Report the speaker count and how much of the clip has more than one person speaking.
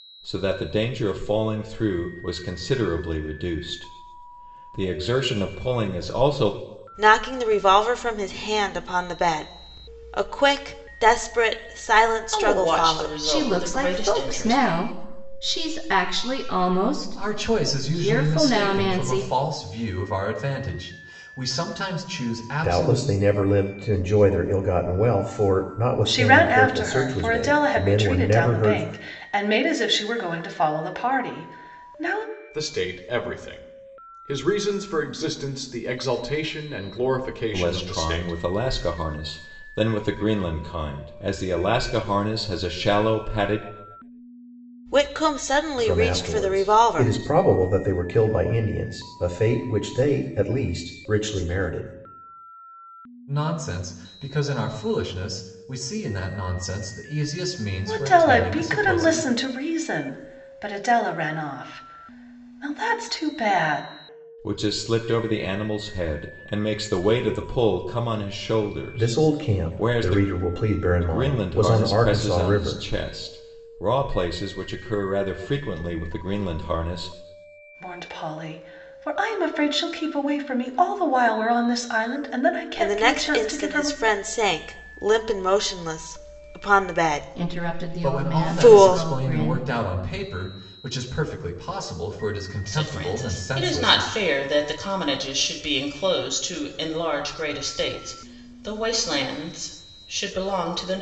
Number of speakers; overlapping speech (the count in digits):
8, about 19%